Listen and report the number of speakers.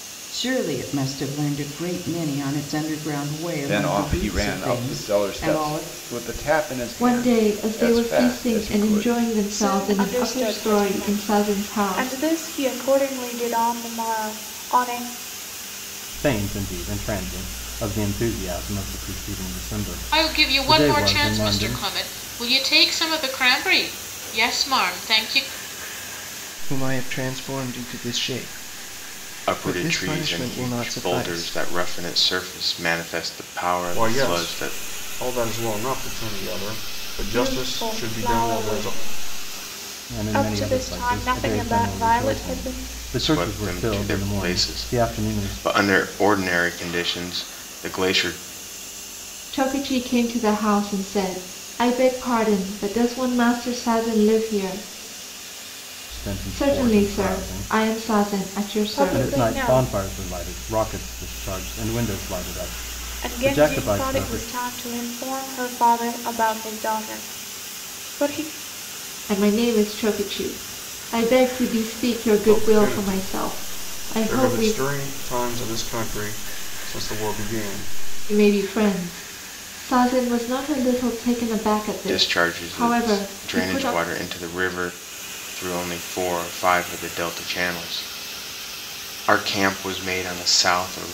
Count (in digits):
9